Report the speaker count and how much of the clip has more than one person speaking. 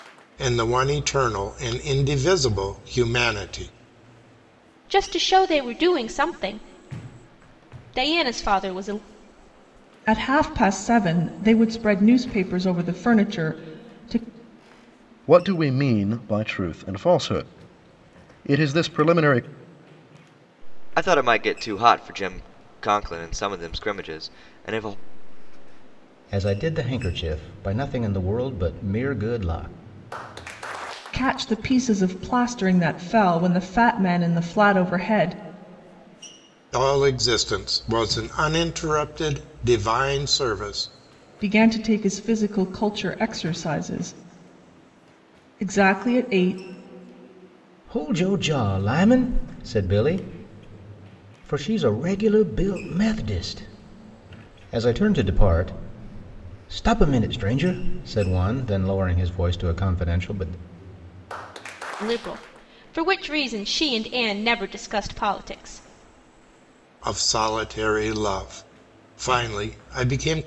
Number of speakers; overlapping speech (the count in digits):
6, no overlap